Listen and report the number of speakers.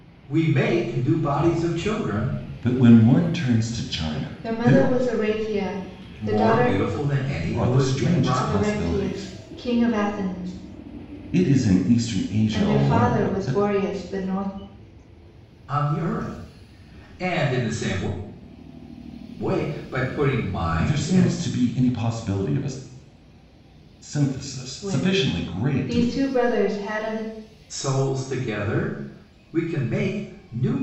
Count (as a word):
three